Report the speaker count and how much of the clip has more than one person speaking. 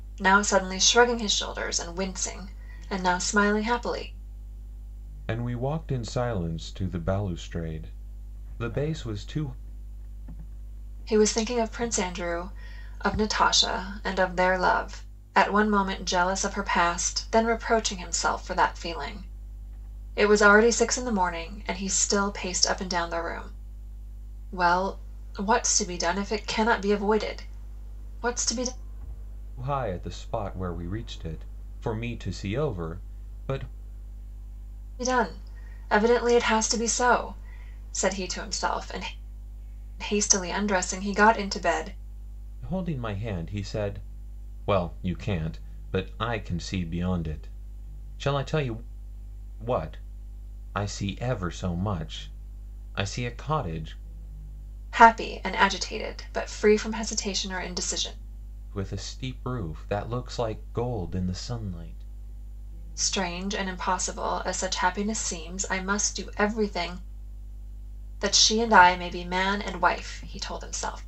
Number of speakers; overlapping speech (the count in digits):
2, no overlap